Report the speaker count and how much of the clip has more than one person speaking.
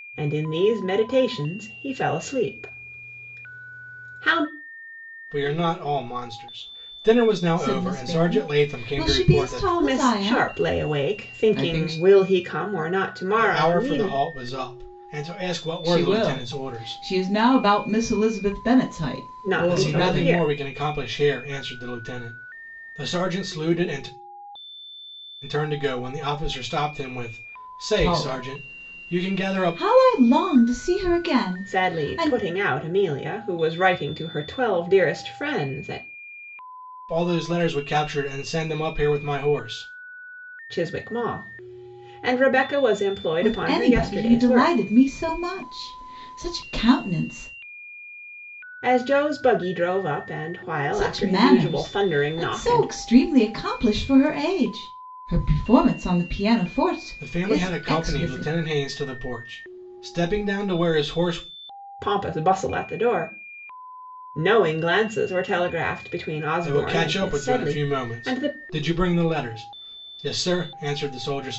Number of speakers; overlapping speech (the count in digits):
3, about 24%